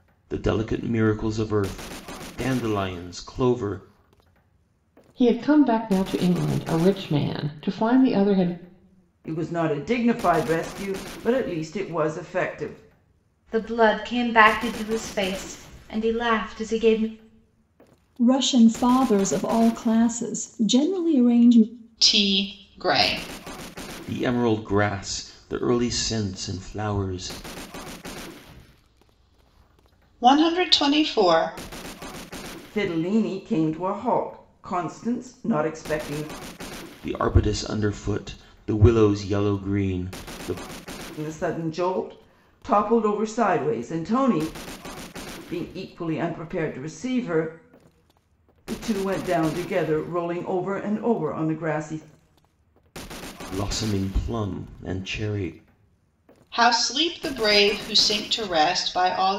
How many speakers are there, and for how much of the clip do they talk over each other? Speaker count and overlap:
6, no overlap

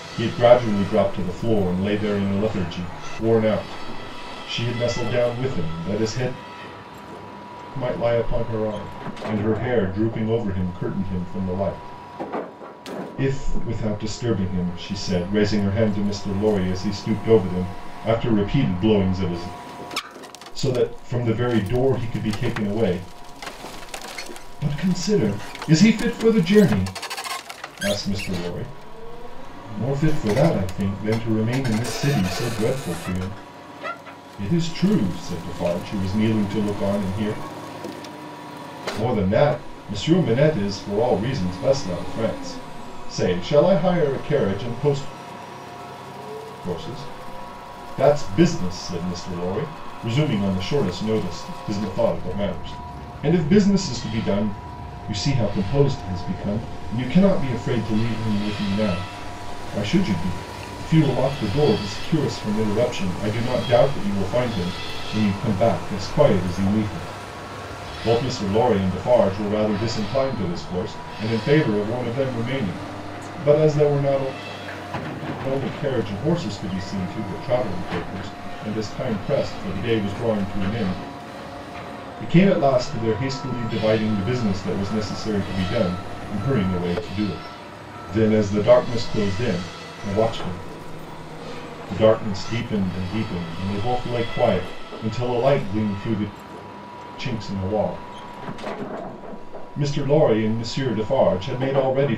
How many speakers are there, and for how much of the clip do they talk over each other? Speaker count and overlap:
1, no overlap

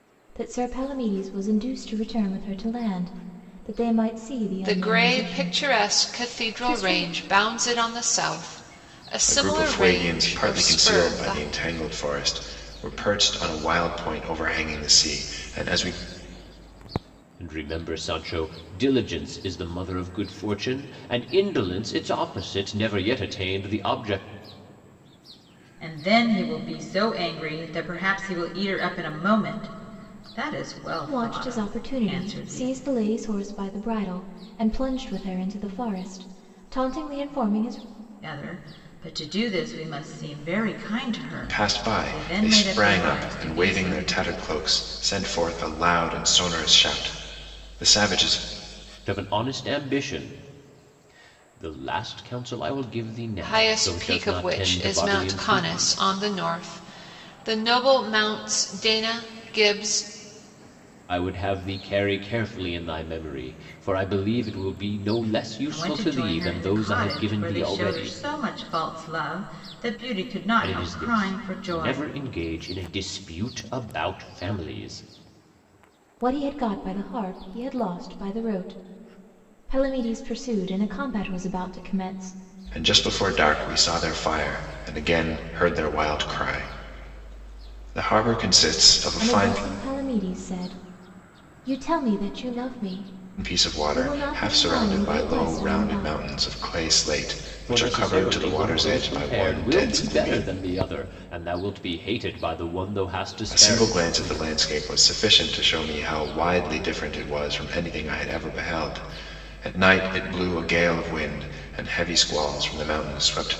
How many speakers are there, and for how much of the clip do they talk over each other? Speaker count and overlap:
5, about 20%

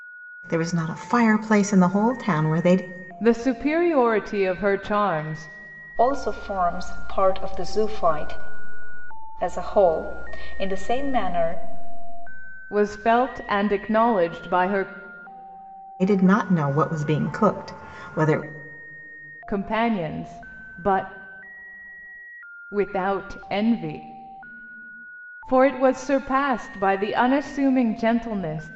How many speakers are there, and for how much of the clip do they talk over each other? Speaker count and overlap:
3, no overlap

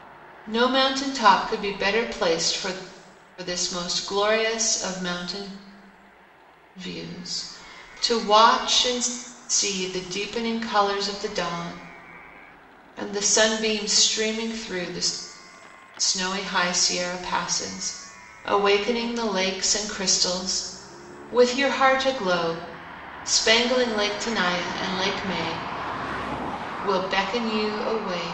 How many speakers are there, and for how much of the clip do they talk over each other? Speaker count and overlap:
1, no overlap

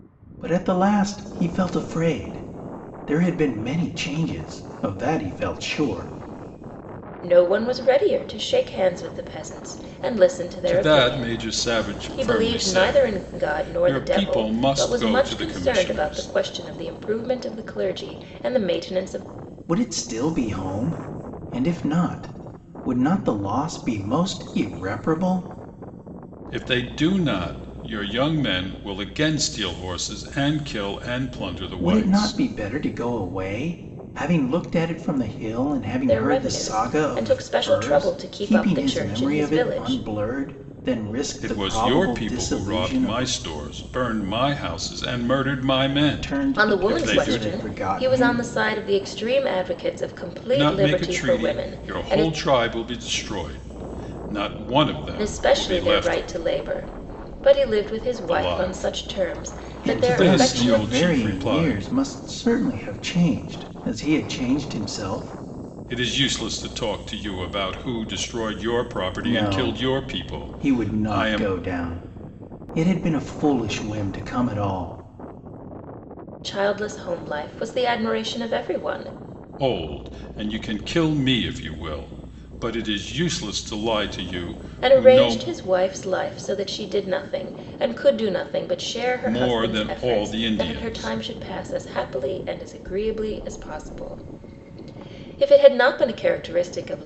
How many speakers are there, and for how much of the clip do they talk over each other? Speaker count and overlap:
3, about 27%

